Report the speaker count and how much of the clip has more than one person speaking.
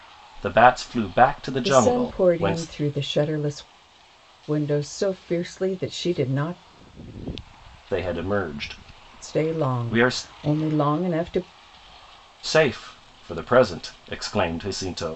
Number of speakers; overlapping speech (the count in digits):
2, about 15%